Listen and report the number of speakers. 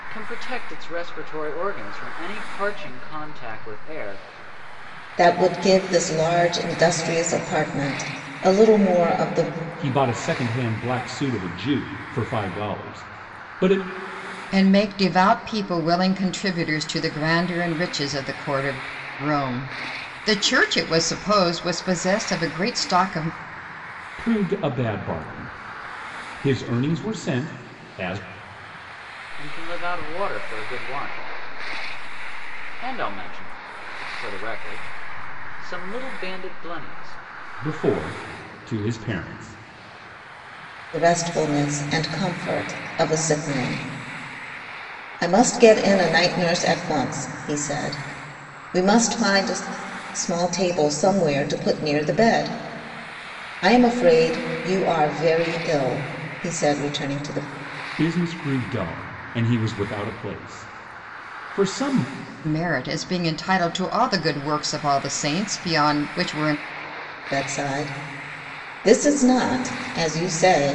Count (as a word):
four